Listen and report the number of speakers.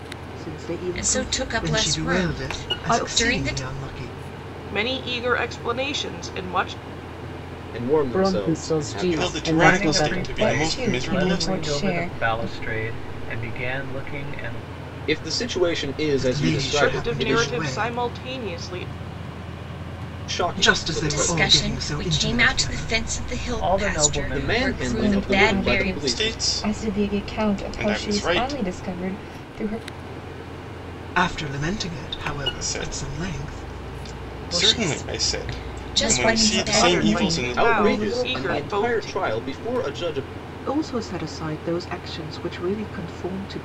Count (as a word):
nine